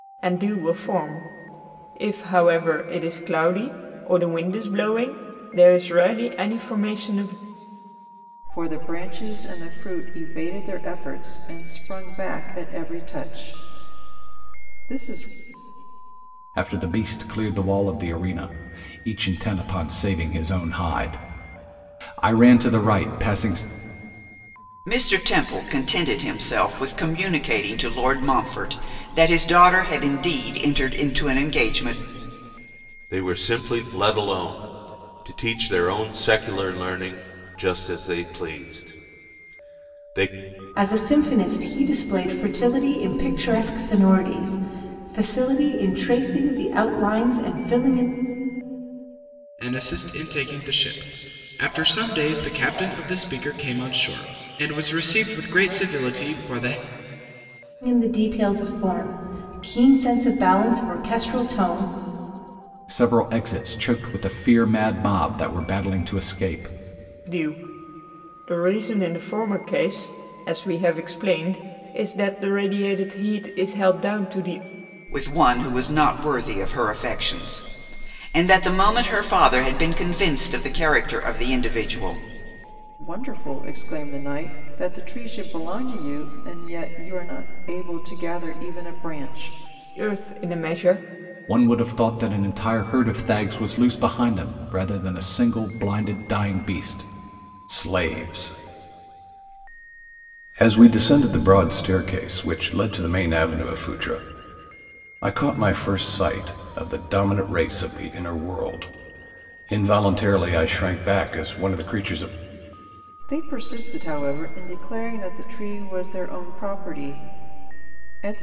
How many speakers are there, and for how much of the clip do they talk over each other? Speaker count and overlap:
7, no overlap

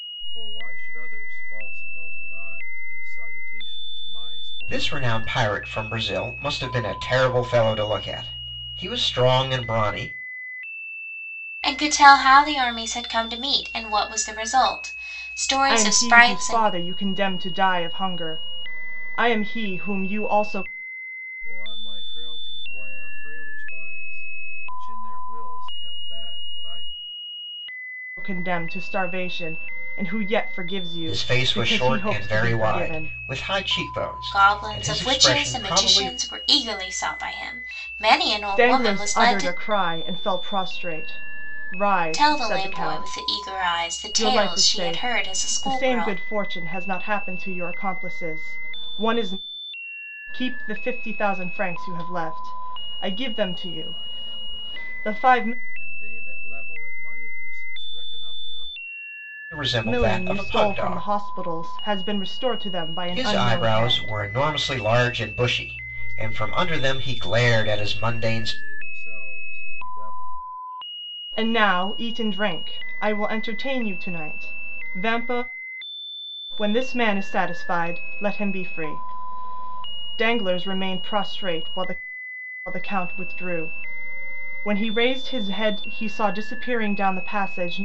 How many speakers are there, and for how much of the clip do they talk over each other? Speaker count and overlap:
4, about 19%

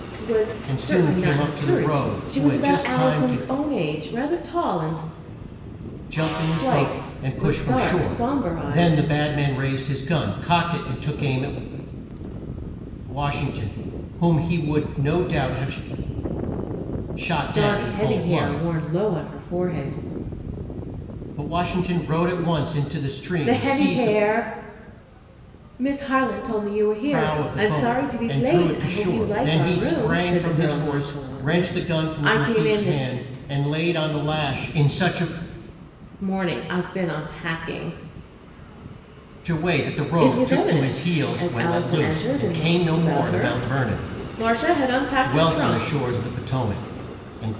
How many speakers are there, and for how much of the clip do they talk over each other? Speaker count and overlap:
2, about 38%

